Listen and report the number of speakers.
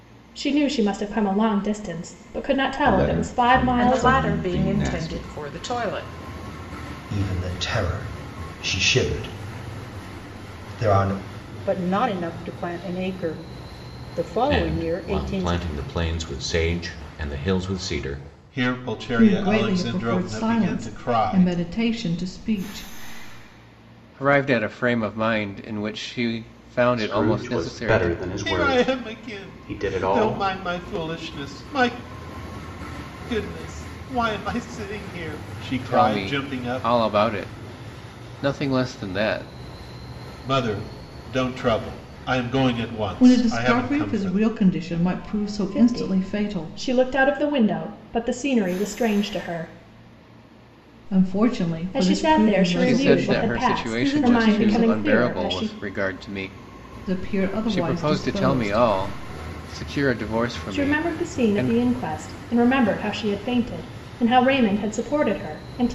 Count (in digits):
10